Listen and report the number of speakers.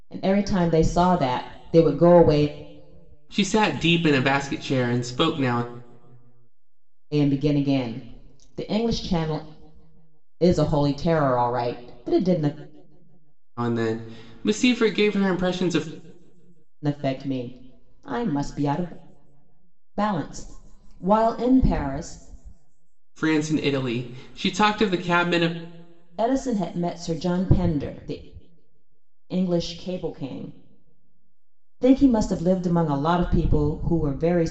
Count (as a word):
two